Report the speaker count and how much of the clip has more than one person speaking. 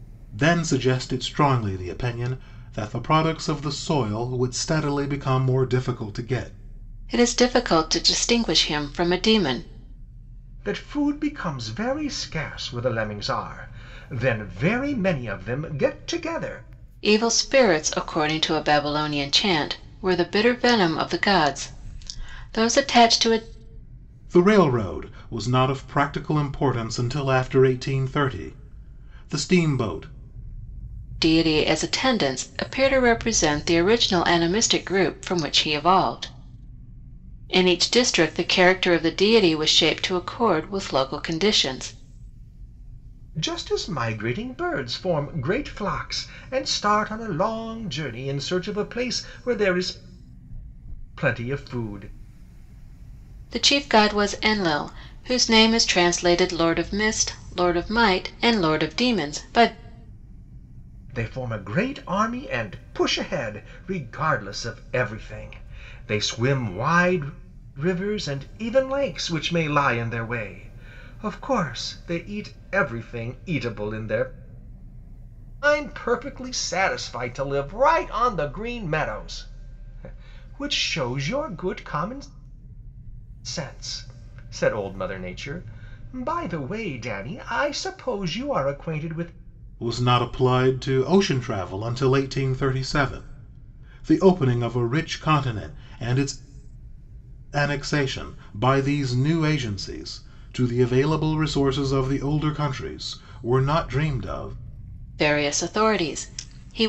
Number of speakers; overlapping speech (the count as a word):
three, no overlap